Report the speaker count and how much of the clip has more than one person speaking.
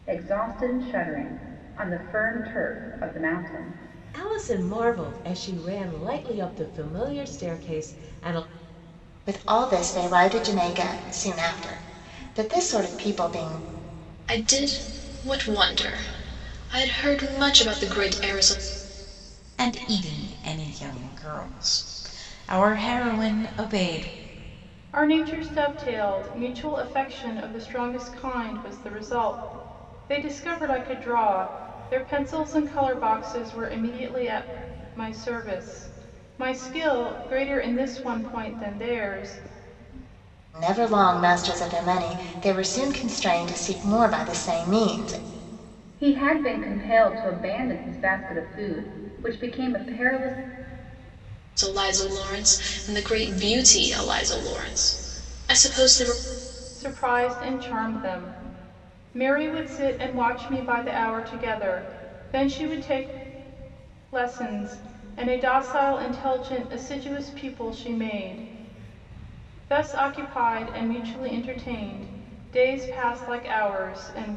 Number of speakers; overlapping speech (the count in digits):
6, no overlap